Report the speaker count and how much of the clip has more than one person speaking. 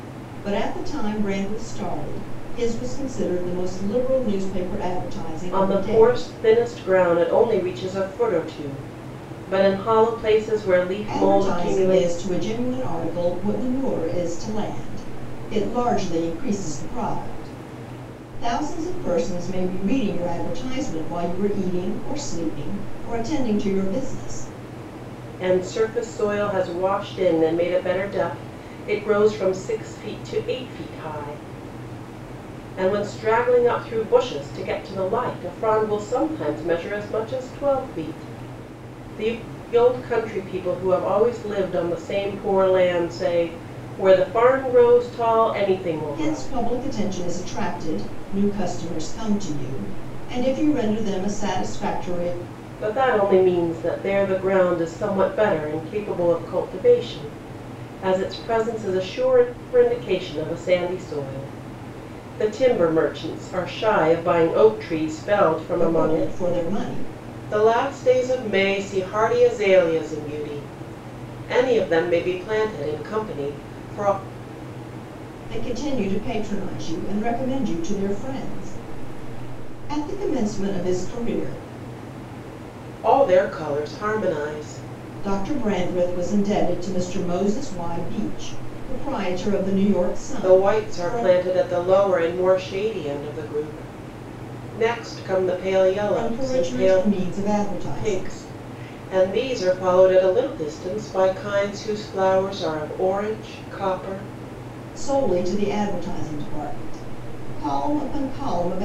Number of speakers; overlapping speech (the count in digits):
2, about 5%